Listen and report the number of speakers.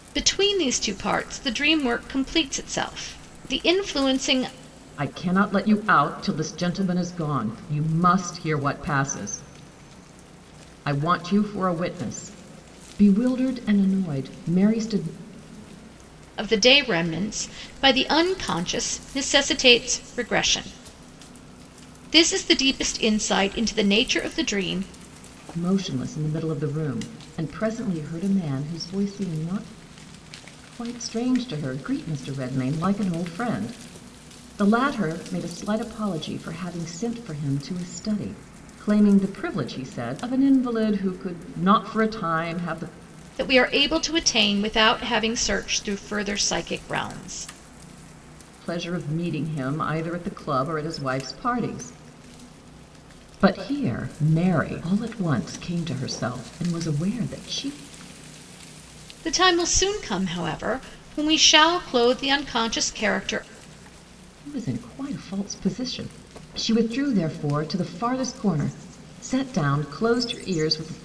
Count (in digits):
2